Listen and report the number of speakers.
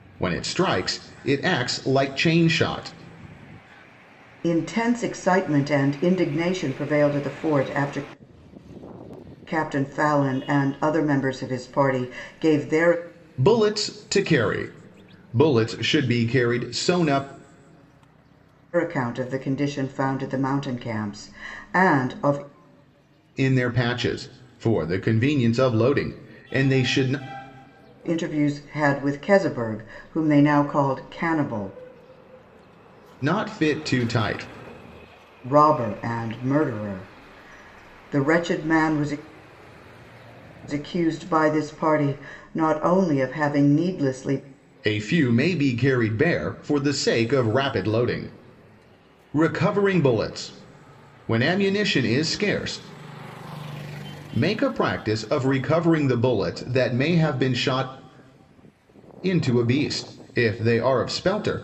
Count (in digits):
2